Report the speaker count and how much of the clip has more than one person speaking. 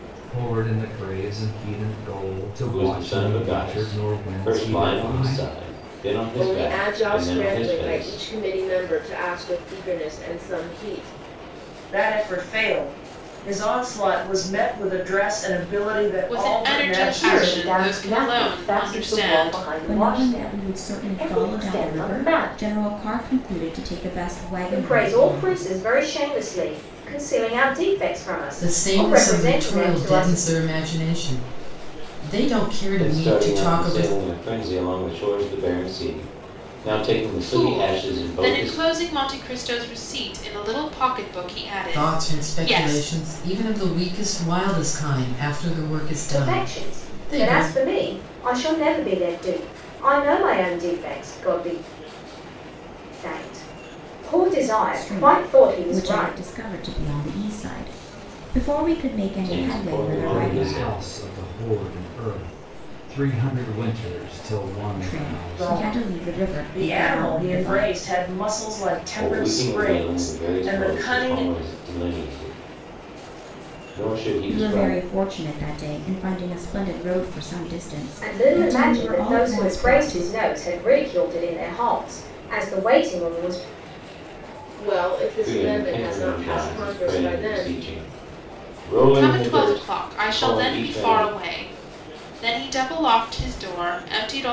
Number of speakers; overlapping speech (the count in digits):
9, about 37%